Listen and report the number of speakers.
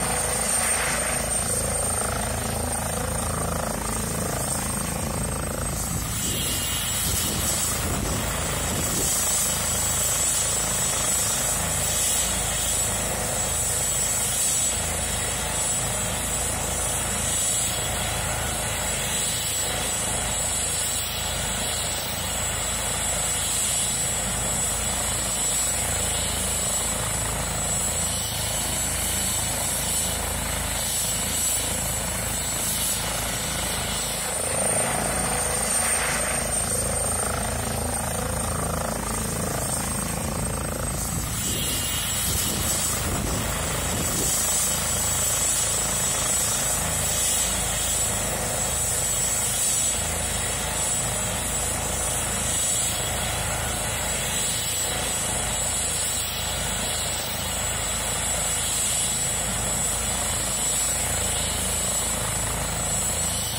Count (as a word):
zero